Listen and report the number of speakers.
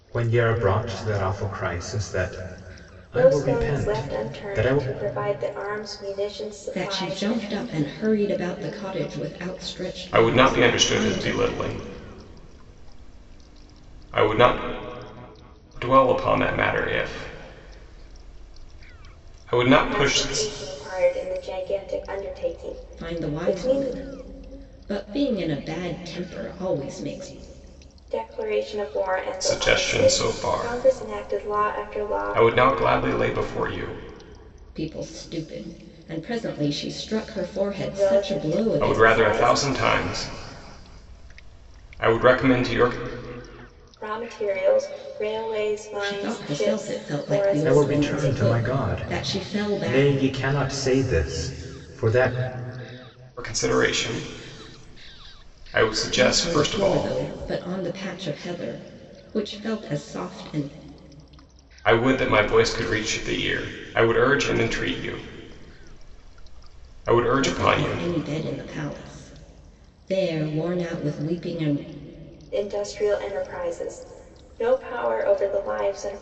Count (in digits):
4